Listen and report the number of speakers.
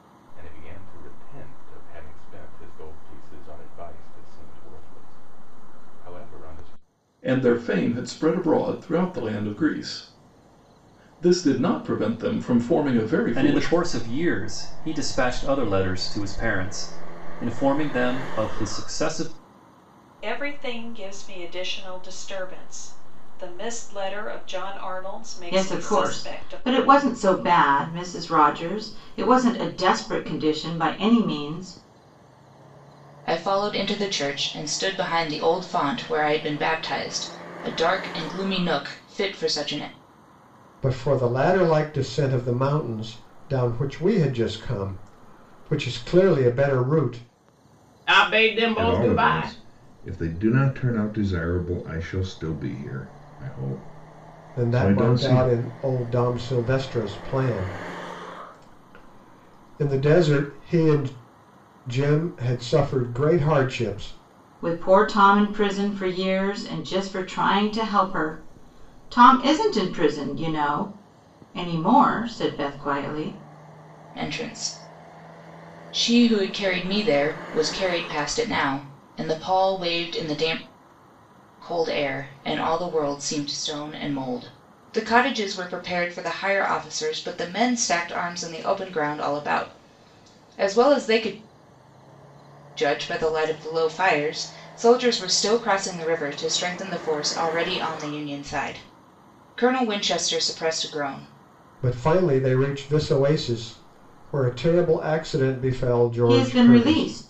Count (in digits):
9